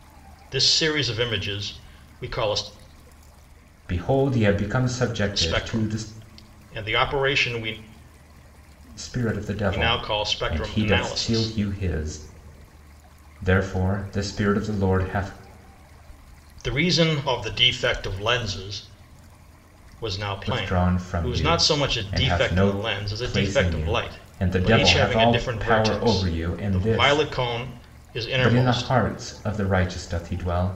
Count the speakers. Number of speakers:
2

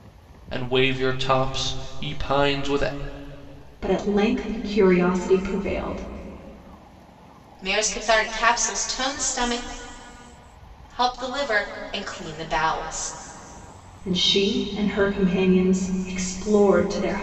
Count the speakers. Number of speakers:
3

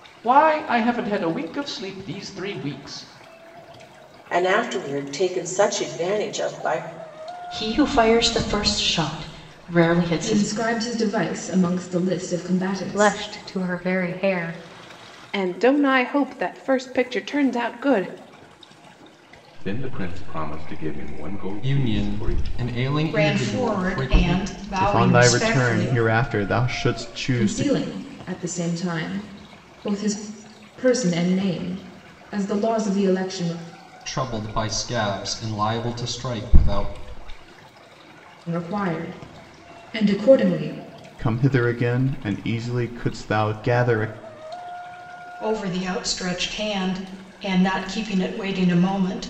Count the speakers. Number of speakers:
10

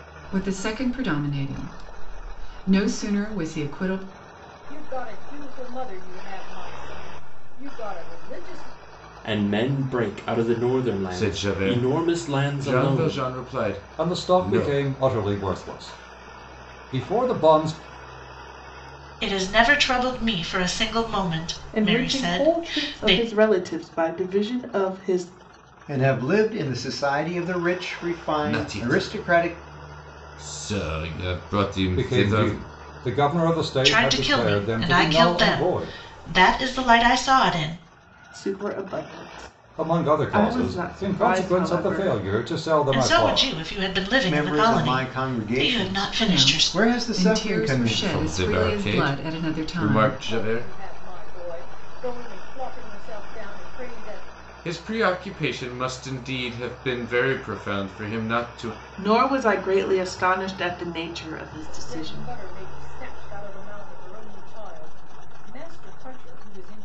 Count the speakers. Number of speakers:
8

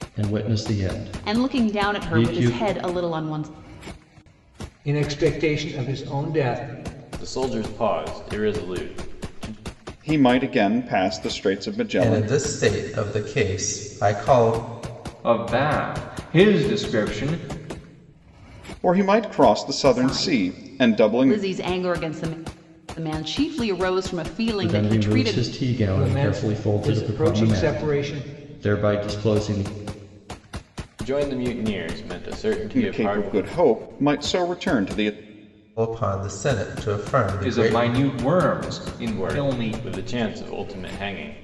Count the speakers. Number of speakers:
7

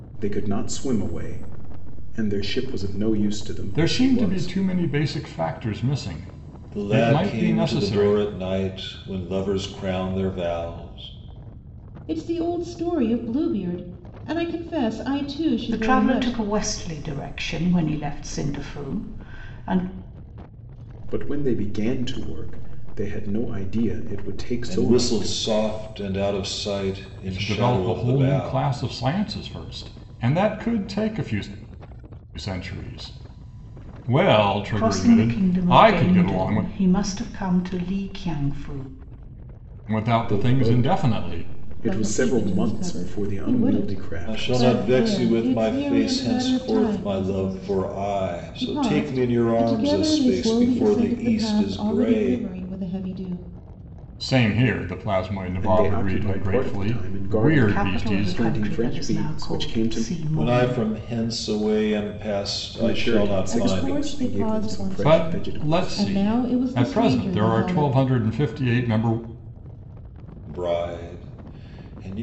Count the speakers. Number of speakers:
5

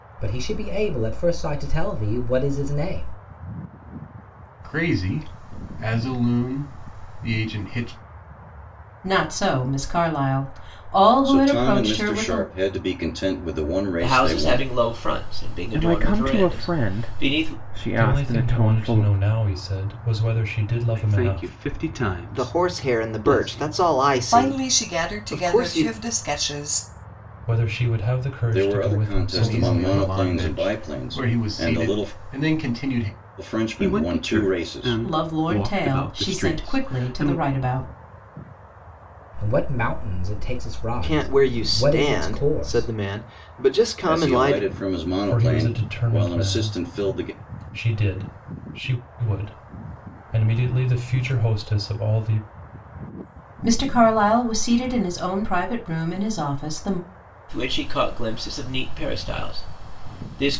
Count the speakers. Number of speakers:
10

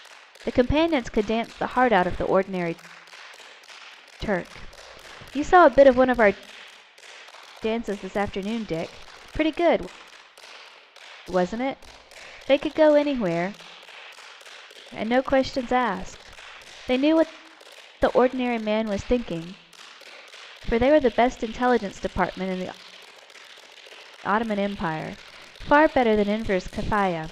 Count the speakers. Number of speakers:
1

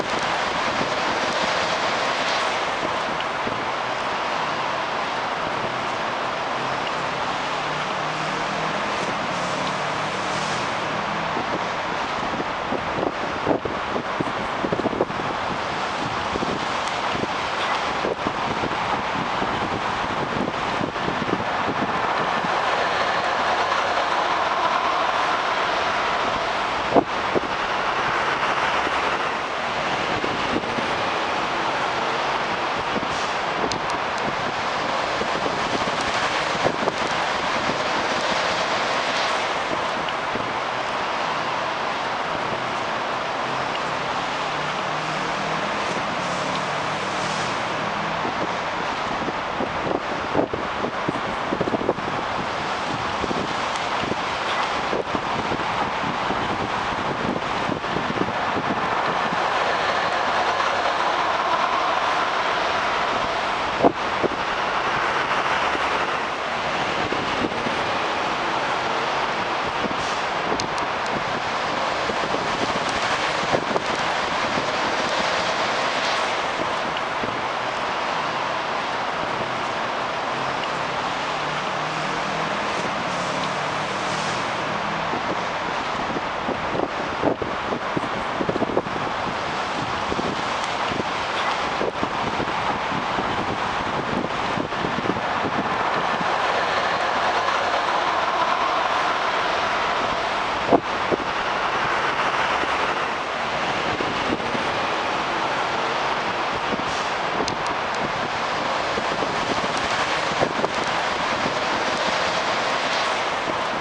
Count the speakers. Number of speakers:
0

